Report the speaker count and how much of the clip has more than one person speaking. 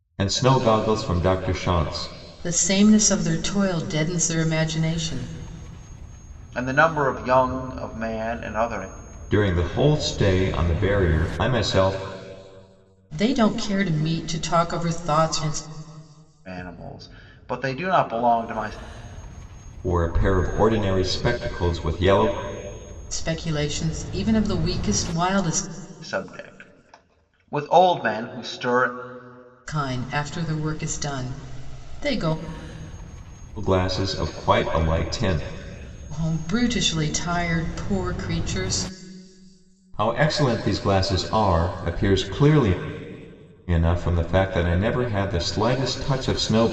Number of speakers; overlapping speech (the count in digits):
3, no overlap